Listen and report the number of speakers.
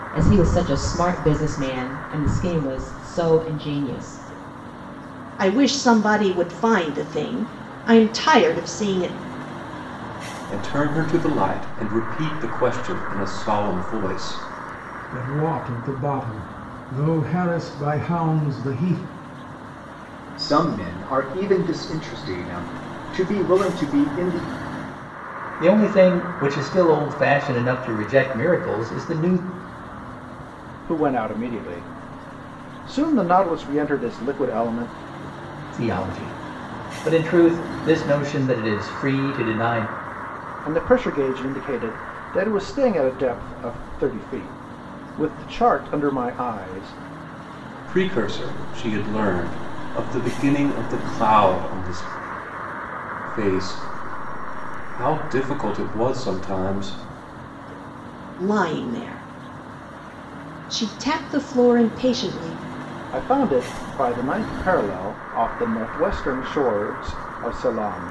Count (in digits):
7